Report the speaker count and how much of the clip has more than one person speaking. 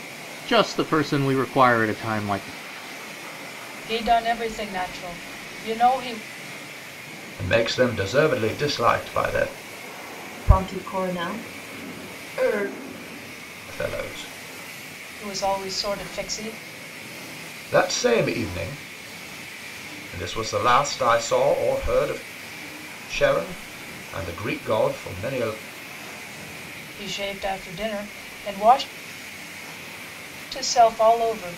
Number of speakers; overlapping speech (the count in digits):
4, no overlap